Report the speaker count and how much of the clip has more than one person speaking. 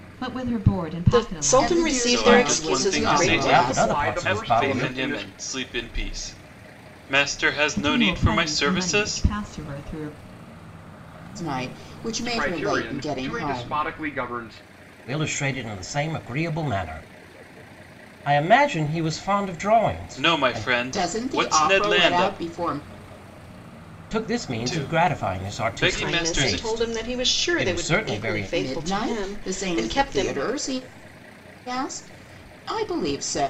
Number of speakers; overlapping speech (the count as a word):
six, about 46%